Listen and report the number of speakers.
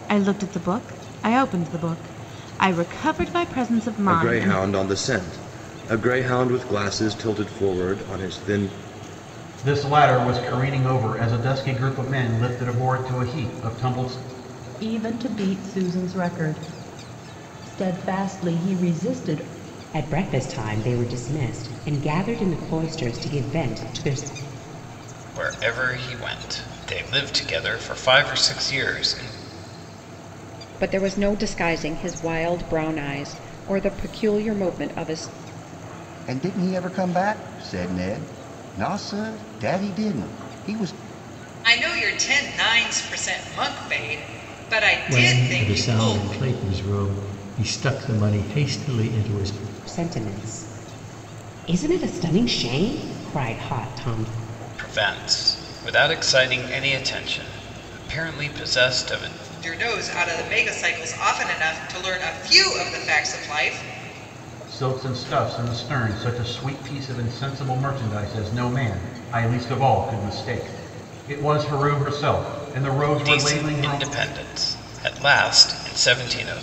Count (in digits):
10